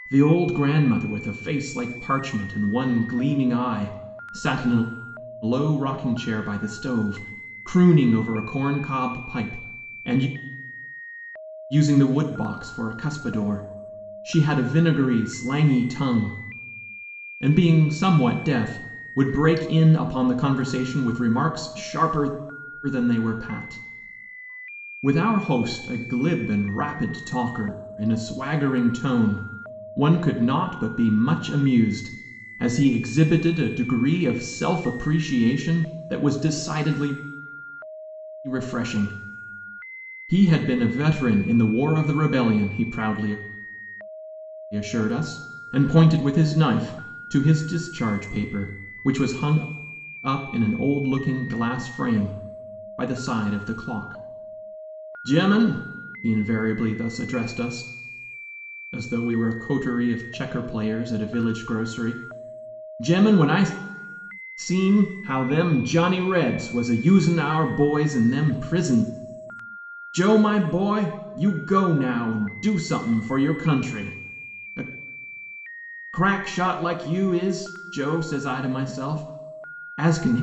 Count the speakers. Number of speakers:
1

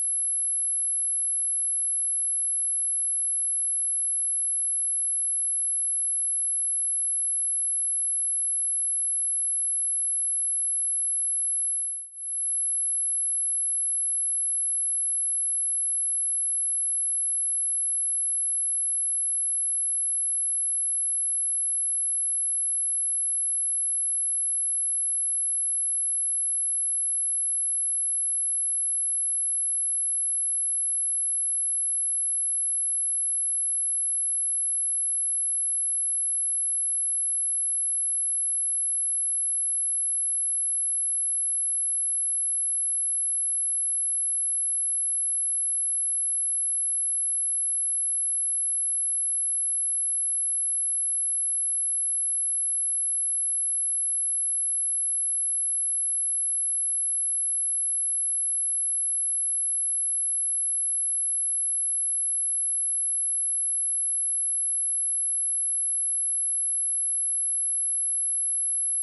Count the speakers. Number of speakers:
0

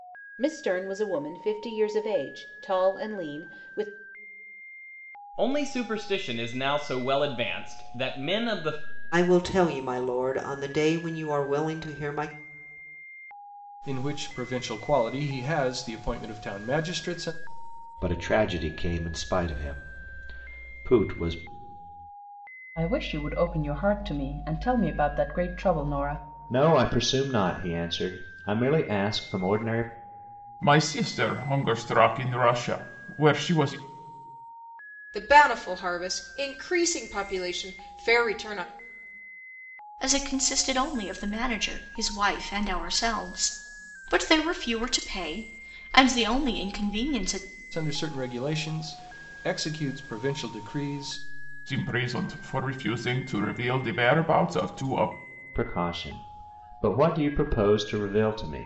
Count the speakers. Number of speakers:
10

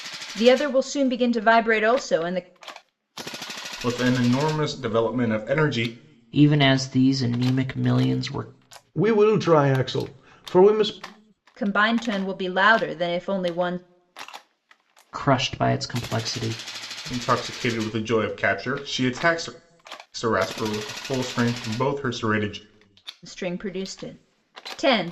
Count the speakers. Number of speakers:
4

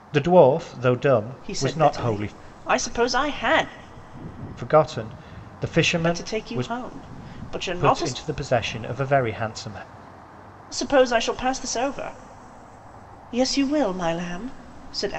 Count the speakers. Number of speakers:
2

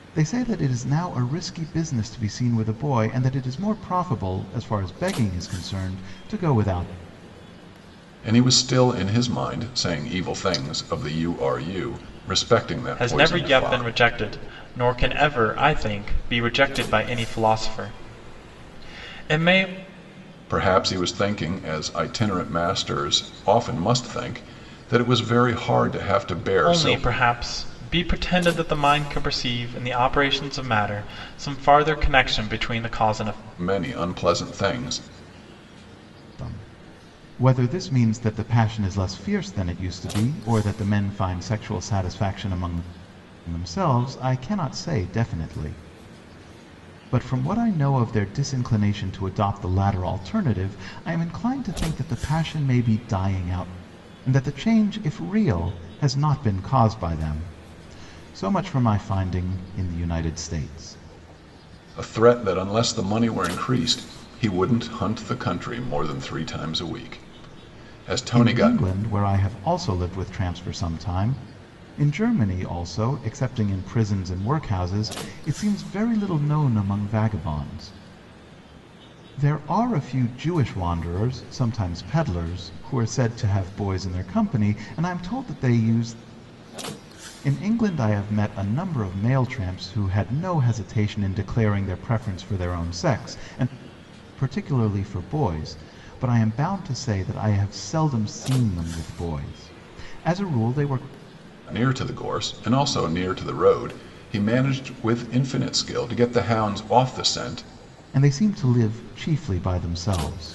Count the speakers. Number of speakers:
3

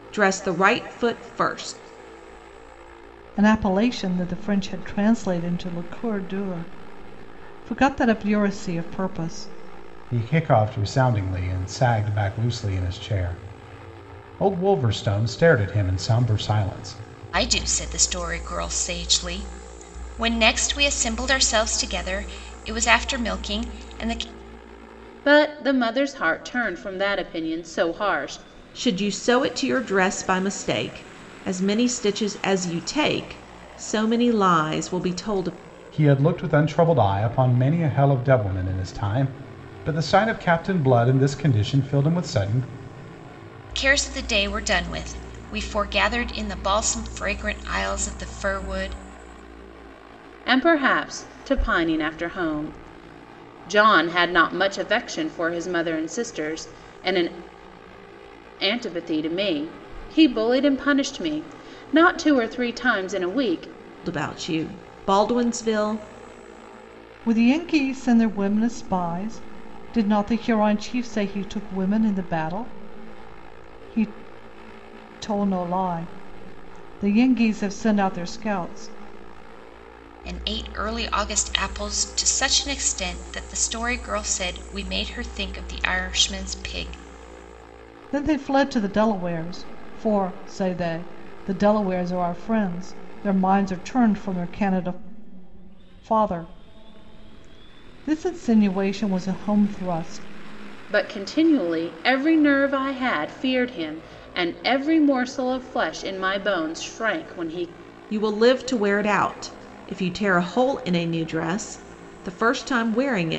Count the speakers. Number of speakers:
5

